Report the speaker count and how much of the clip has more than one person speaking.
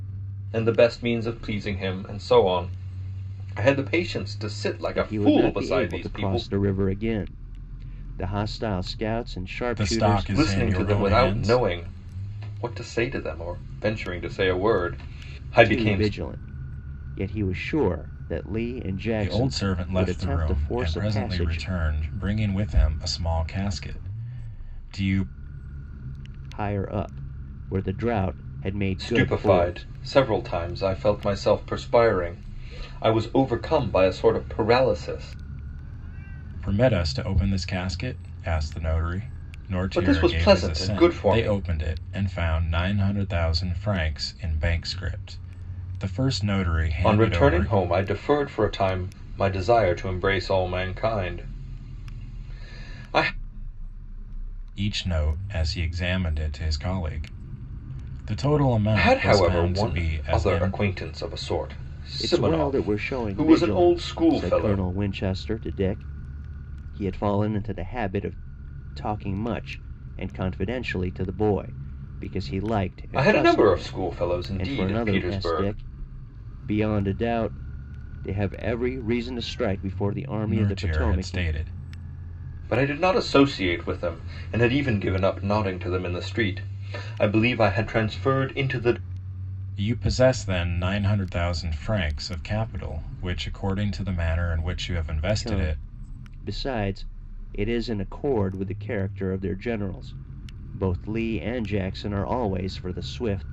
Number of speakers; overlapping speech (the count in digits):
3, about 18%